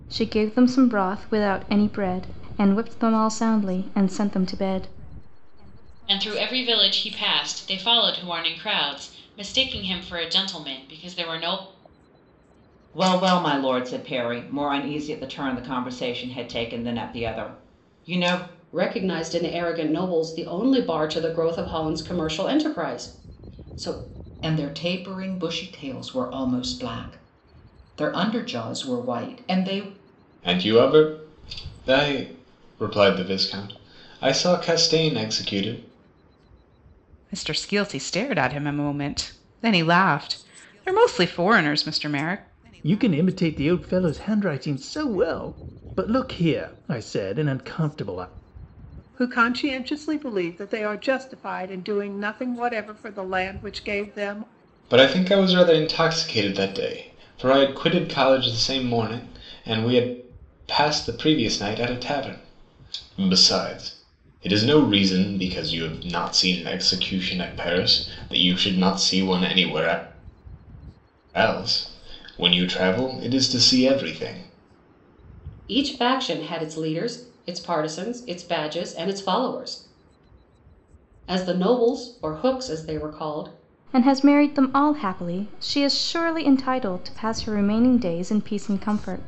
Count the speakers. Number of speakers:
9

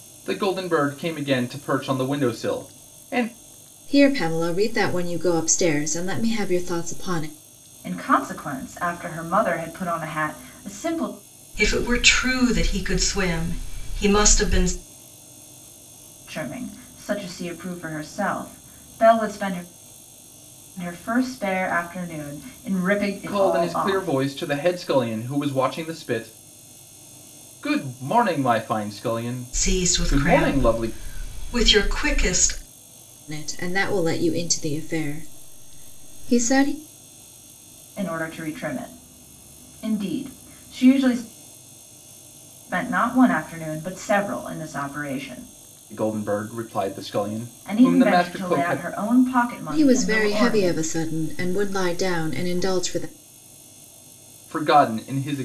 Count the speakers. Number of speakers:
4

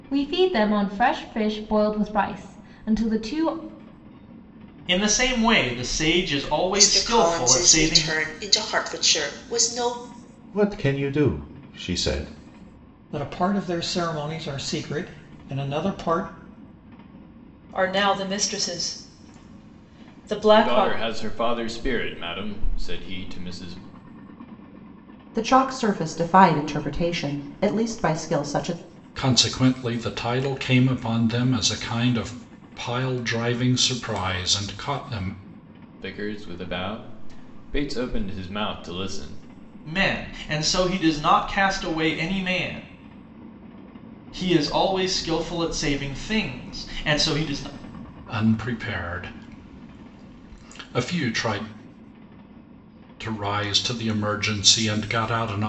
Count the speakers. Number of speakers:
9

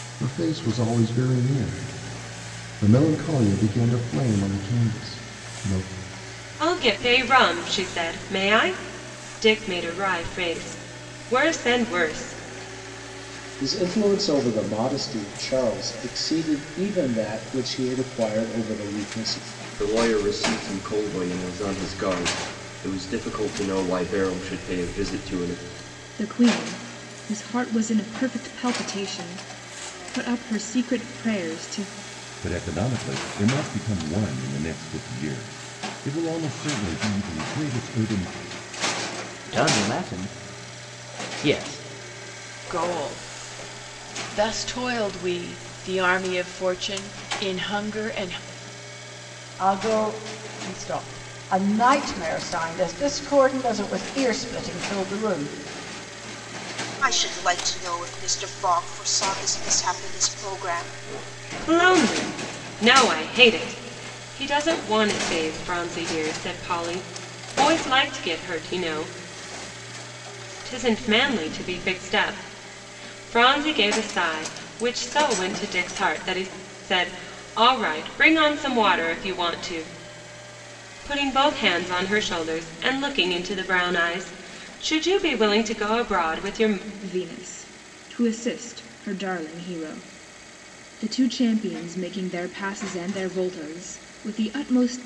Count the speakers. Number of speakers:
10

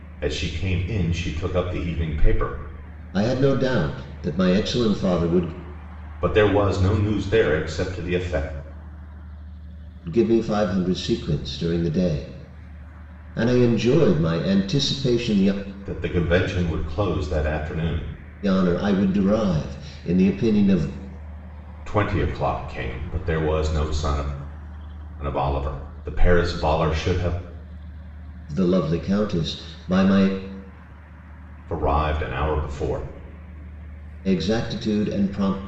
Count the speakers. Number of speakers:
2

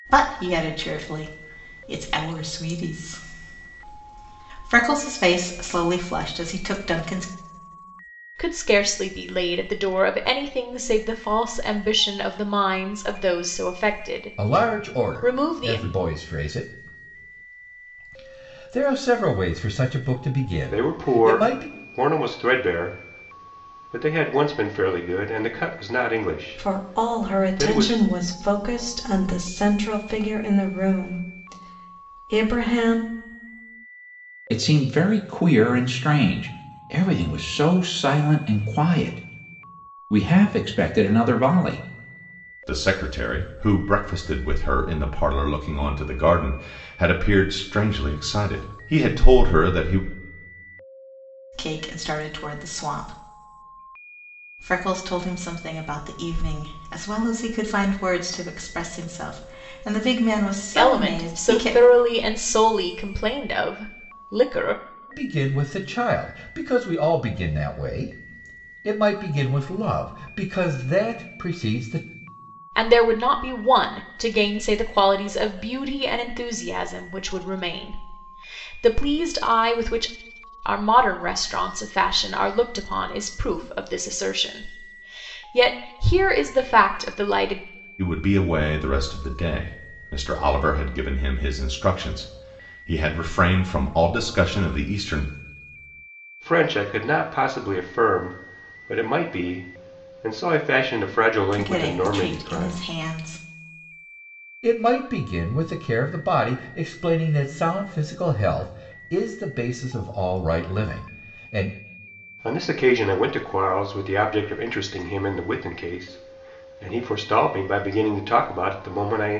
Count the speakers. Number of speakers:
7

